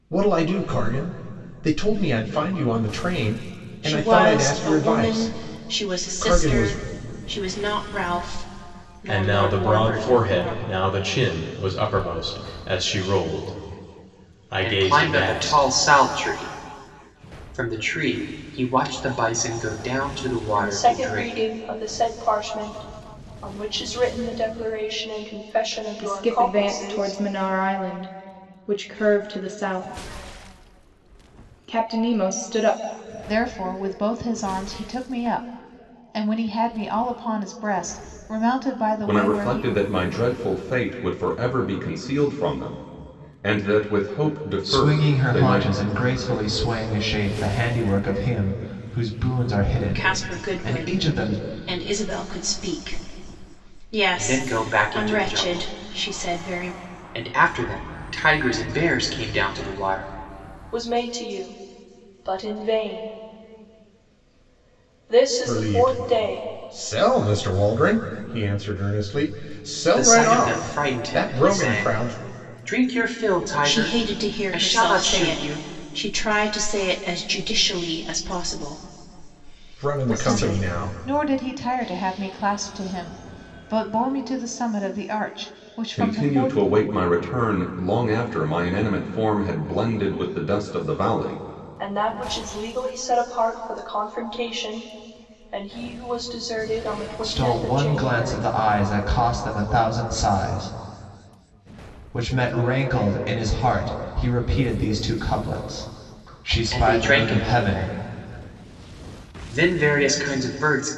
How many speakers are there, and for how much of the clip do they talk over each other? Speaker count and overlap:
nine, about 21%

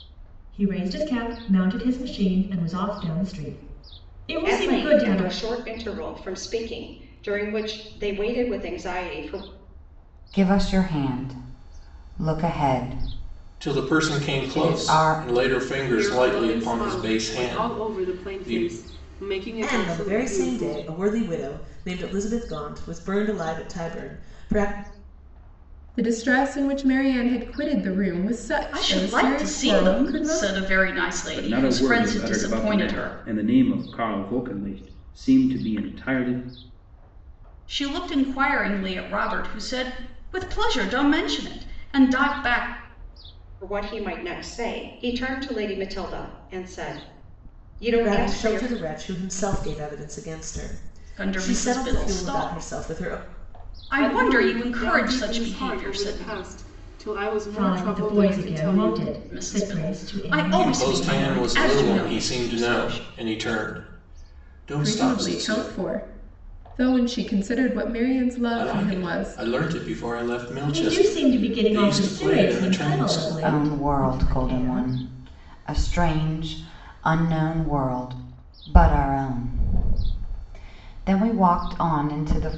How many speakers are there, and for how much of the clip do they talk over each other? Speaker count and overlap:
nine, about 33%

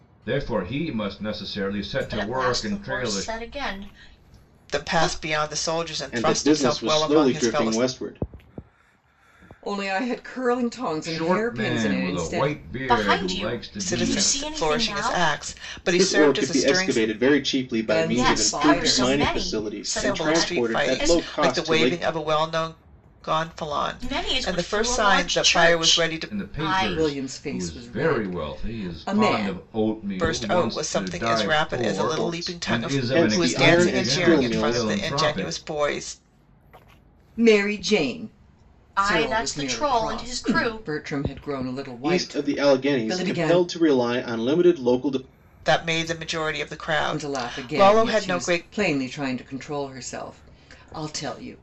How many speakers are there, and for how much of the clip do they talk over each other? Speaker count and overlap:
five, about 56%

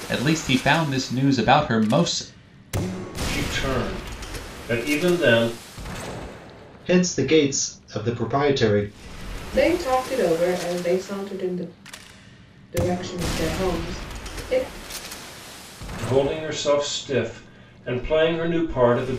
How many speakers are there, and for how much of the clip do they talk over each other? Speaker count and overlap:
four, no overlap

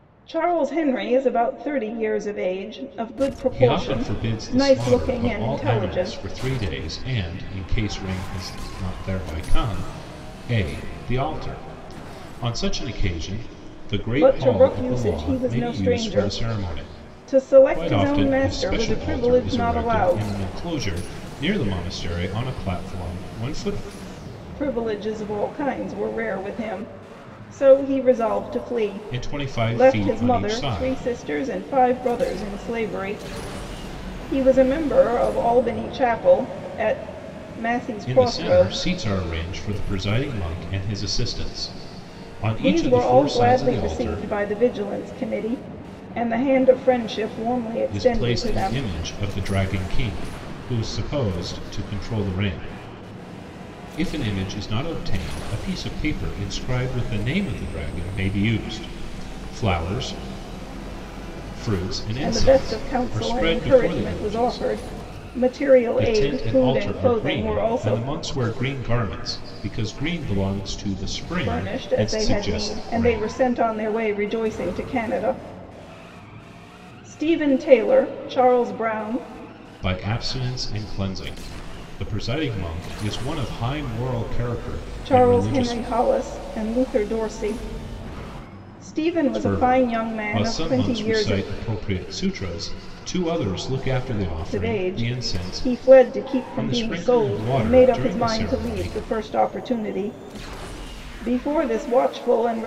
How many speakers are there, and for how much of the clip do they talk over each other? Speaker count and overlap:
two, about 26%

